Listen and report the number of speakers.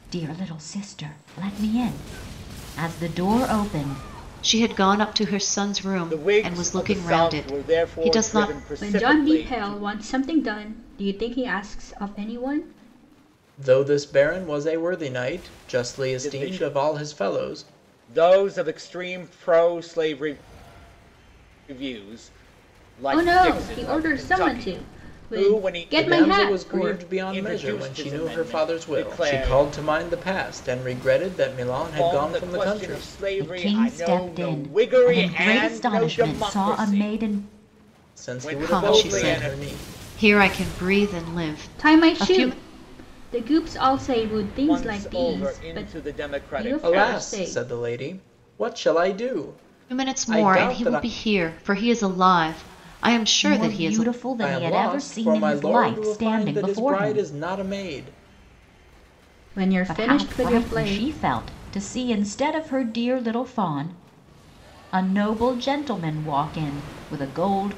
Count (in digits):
5